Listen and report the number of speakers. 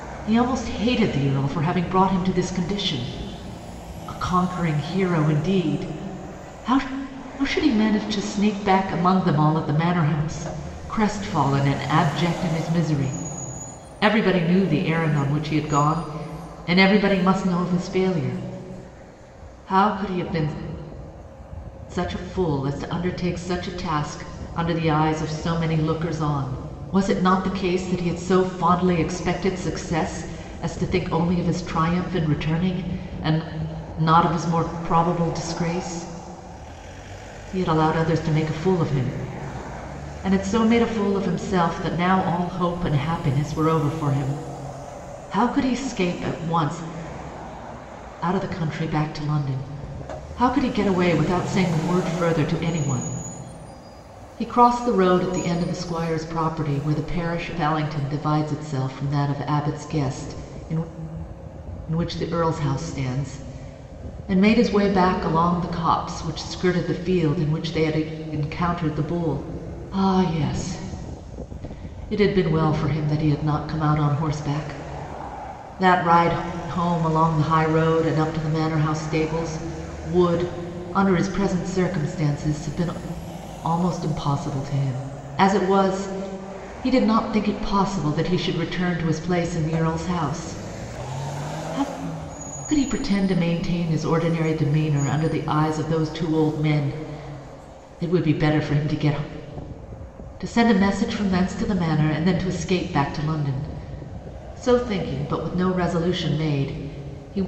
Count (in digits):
1